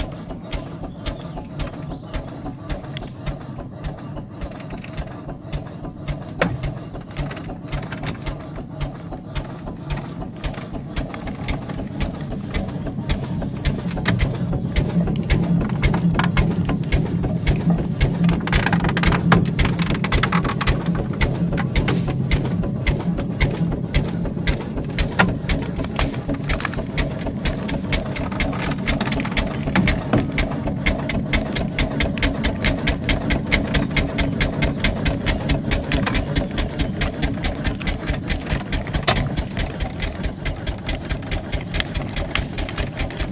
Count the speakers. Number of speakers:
0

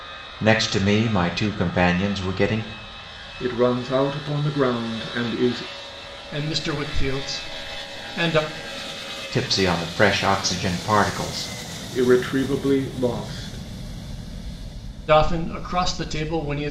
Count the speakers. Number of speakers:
3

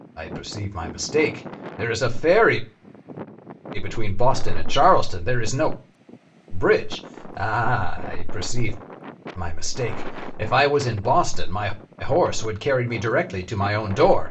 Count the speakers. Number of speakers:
1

